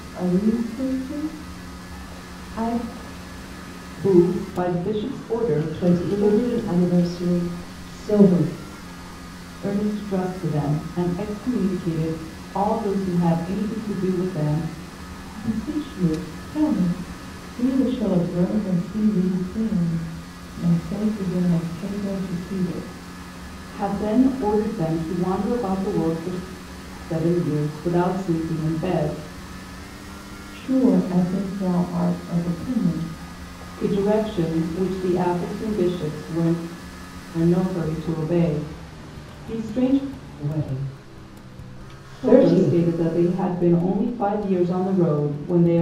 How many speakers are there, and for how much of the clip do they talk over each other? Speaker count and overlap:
3, about 4%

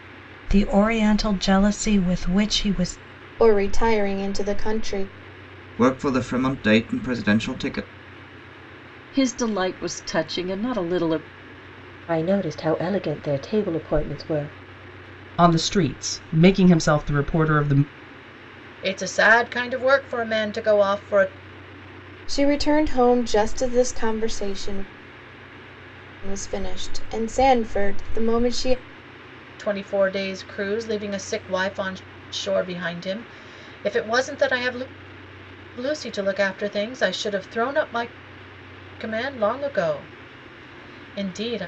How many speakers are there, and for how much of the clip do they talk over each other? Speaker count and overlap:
7, no overlap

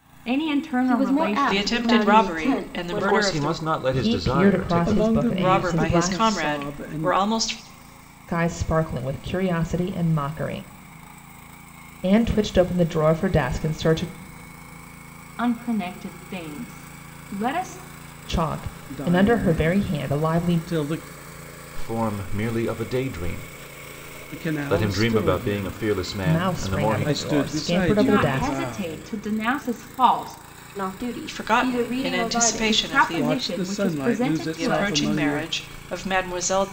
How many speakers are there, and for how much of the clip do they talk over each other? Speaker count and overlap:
6, about 43%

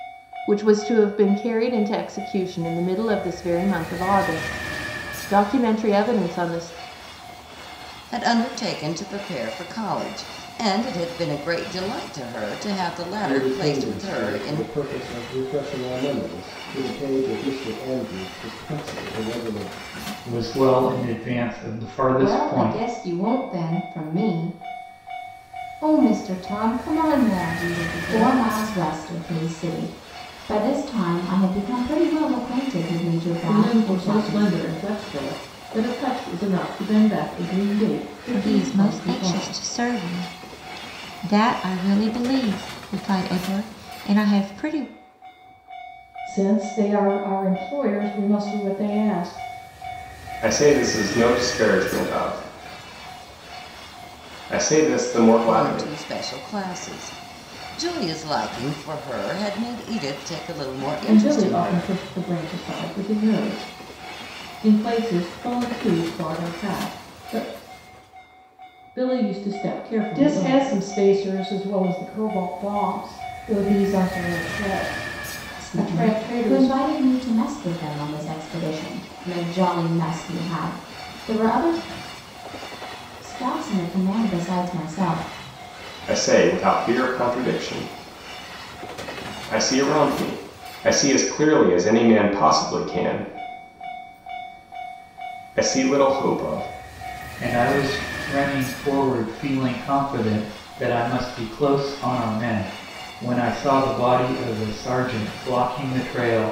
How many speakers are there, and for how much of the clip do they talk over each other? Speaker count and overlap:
10, about 8%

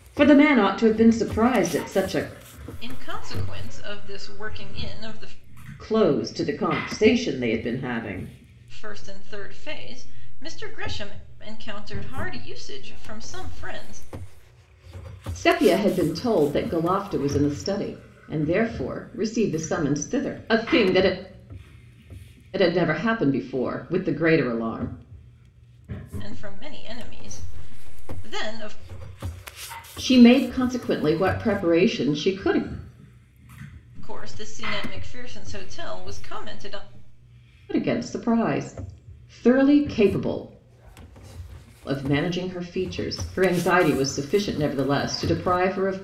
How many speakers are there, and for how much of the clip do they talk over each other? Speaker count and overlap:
2, no overlap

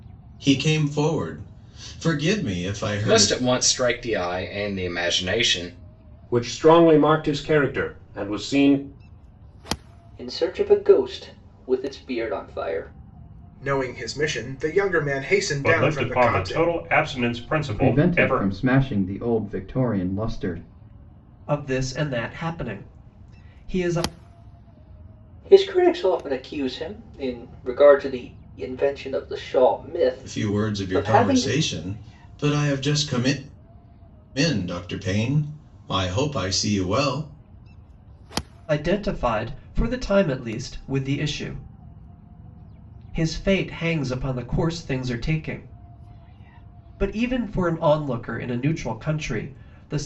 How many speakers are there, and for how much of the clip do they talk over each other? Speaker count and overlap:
8, about 7%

